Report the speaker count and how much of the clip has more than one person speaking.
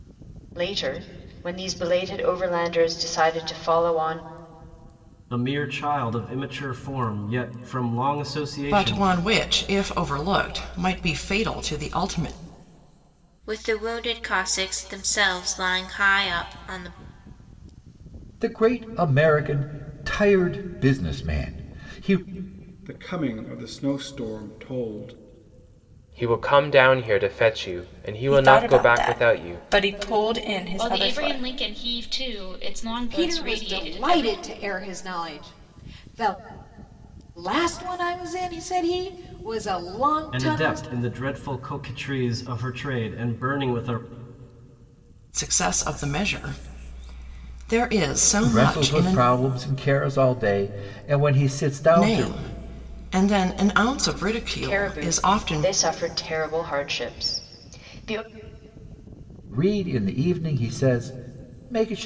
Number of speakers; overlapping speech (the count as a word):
ten, about 11%